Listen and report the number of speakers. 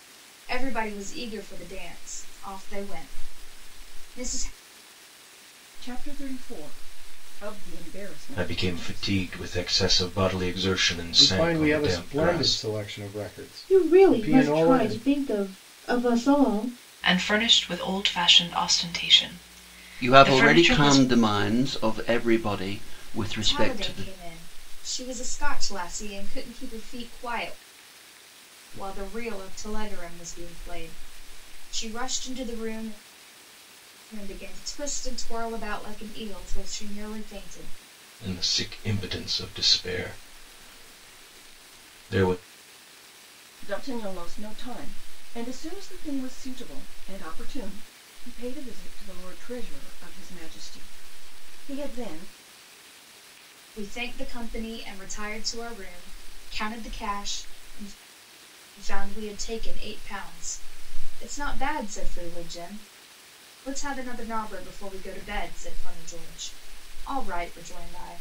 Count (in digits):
7